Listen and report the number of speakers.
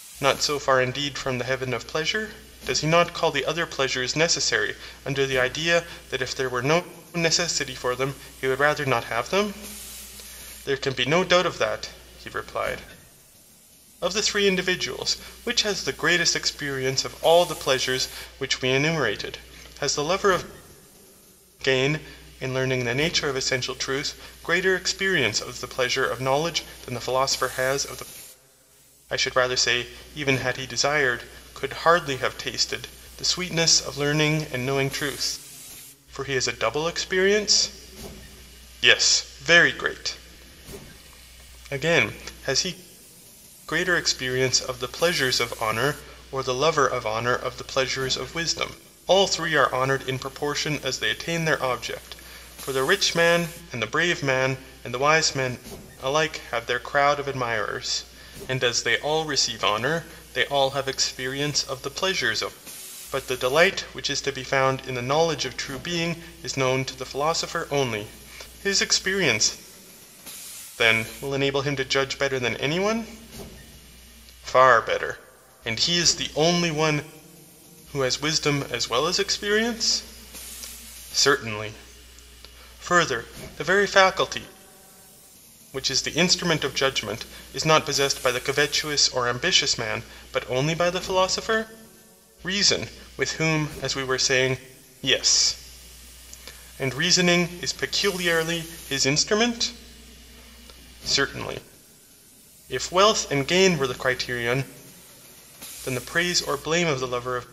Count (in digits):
1